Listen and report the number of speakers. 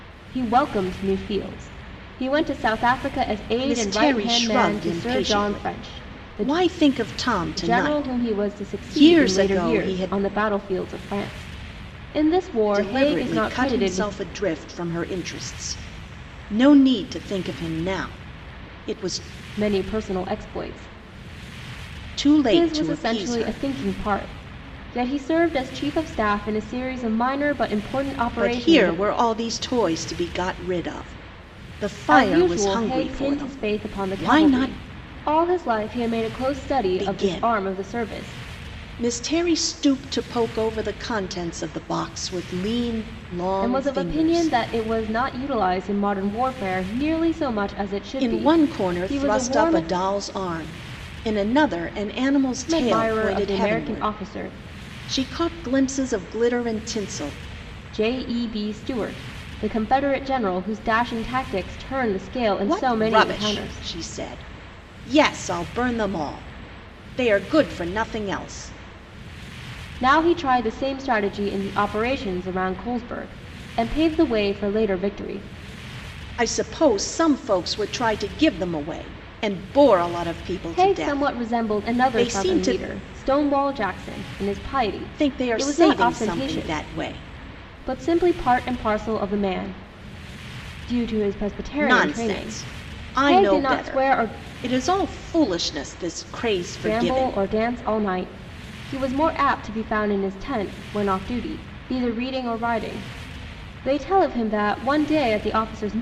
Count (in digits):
2